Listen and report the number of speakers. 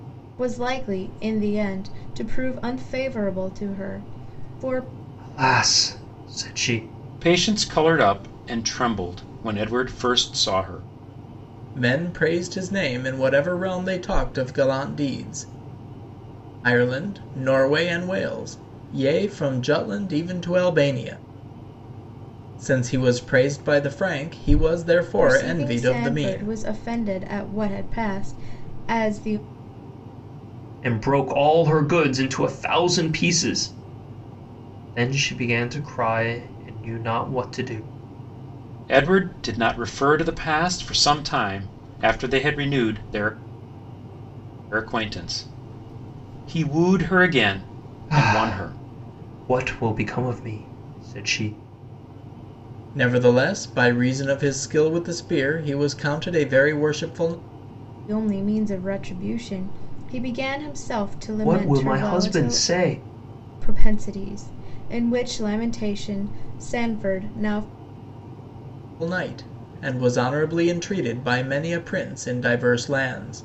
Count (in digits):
4